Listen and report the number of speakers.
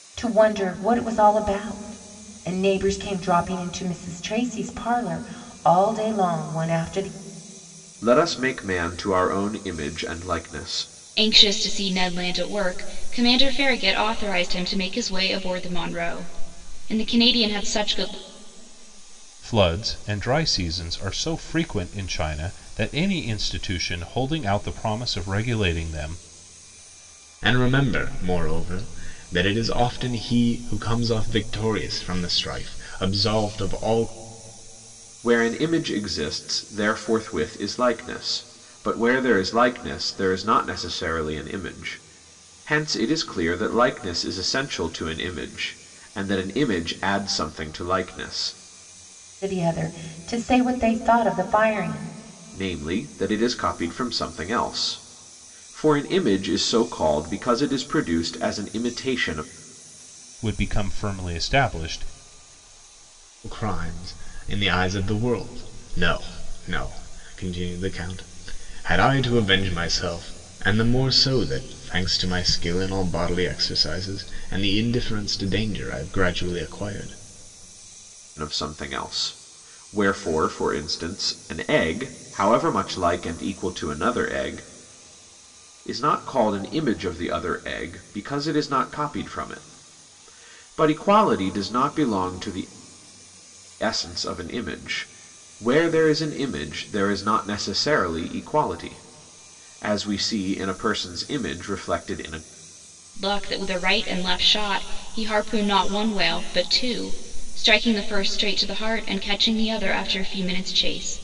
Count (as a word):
five